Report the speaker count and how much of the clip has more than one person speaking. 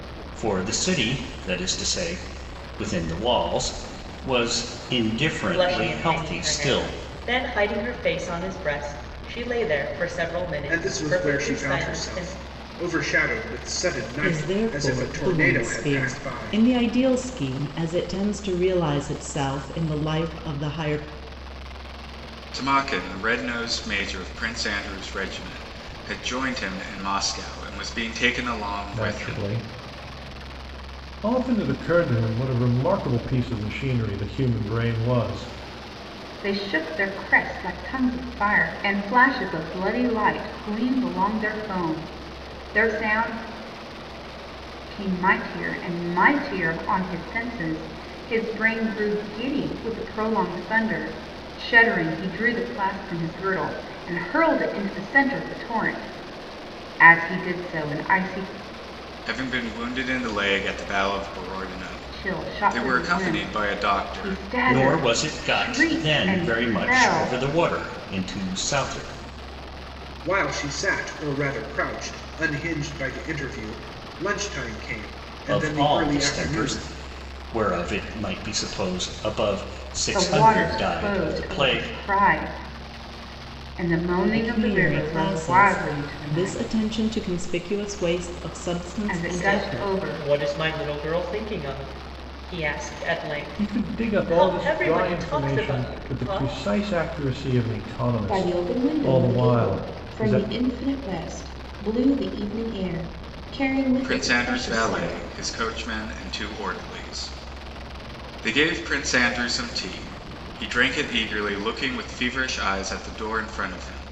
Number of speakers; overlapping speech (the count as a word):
seven, about 22%